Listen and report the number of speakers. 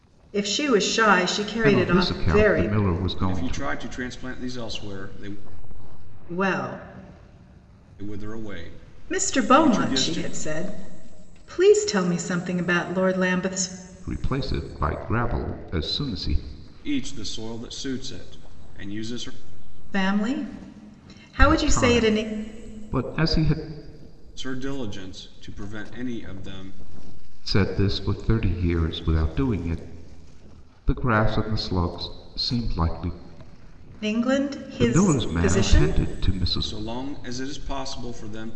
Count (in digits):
3